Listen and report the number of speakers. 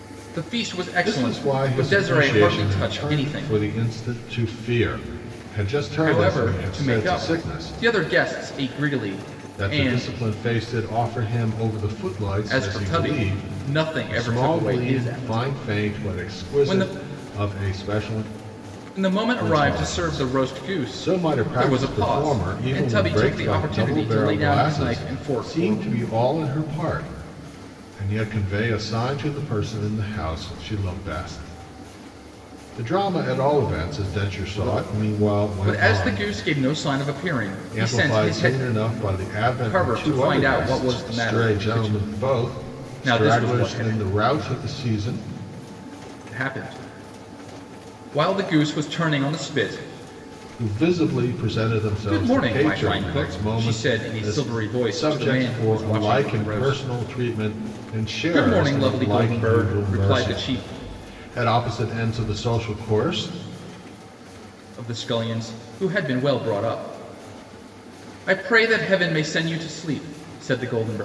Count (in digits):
2